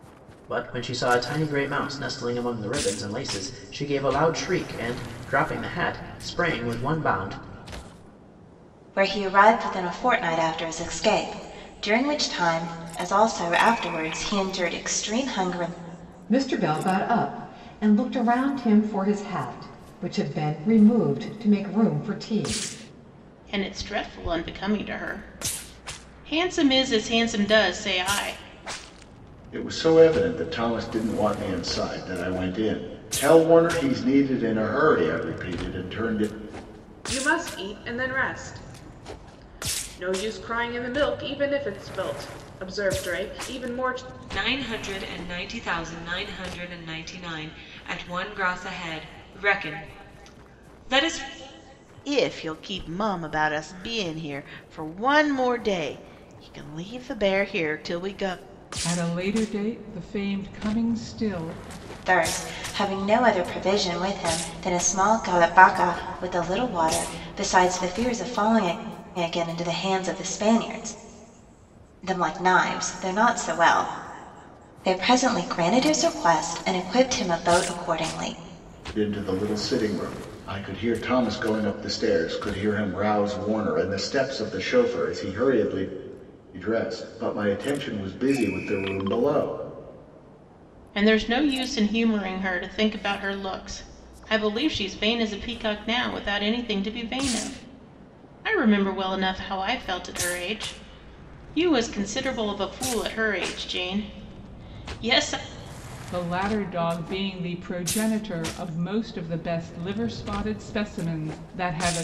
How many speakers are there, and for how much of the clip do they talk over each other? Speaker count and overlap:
9, no overlap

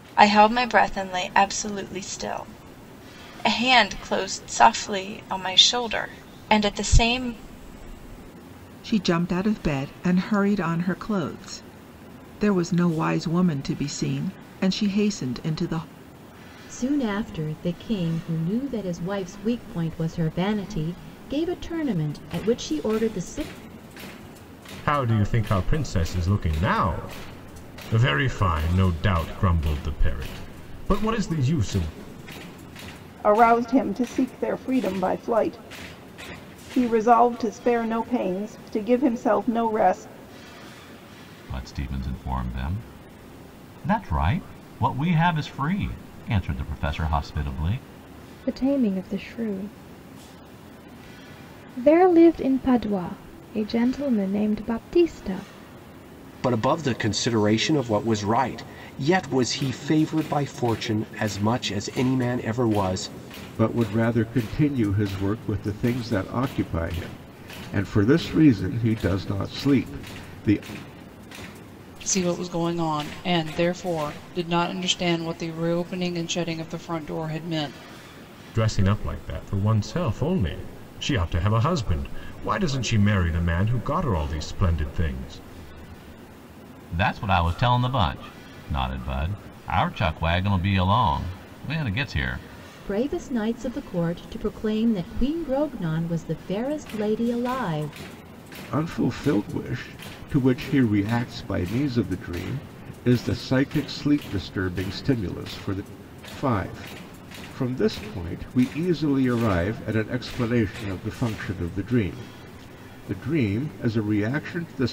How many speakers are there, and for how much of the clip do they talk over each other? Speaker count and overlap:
10, no overlap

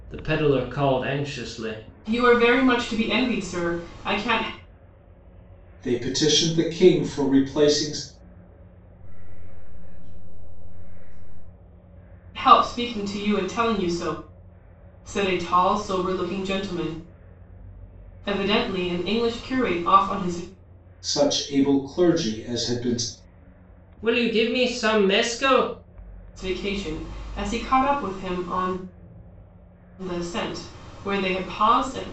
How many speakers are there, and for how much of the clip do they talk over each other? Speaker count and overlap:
4, no overlap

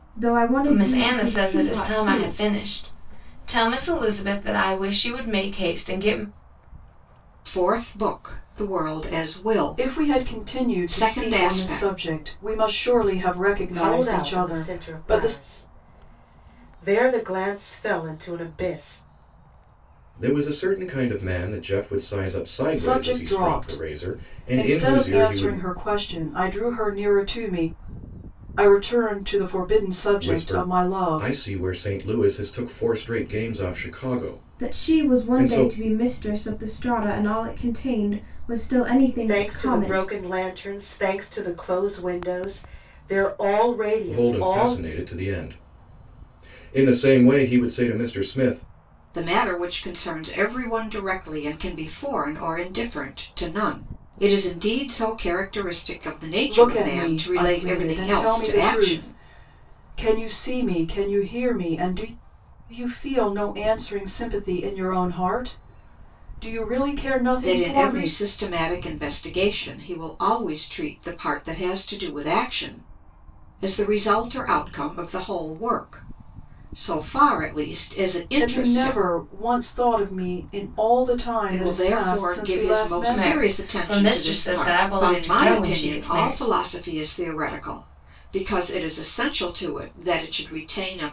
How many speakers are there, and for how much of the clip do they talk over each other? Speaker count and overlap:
6, about 24%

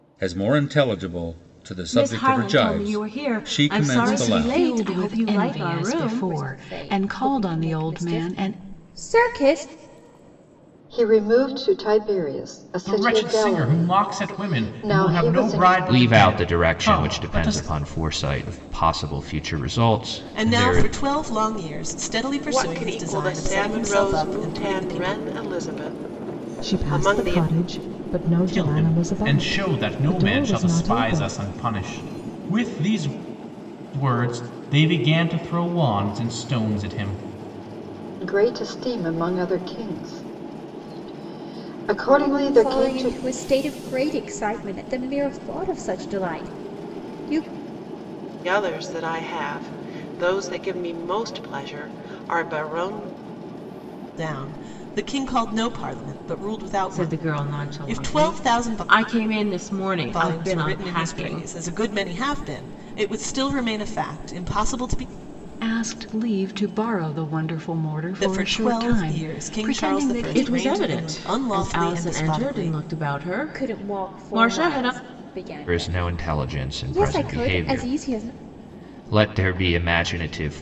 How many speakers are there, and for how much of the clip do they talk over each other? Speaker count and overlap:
10, about 39%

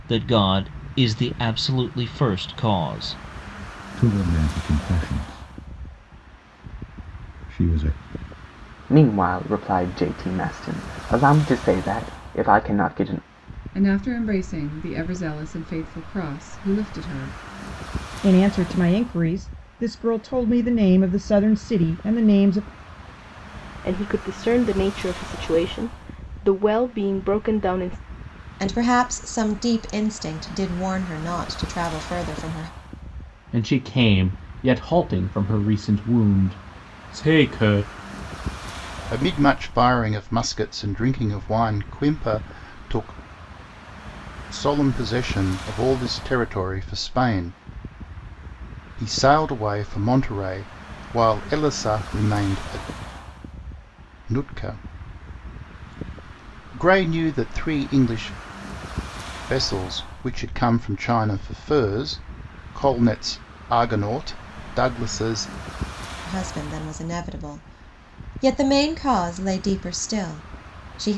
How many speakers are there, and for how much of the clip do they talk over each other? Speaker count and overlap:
9, no overlap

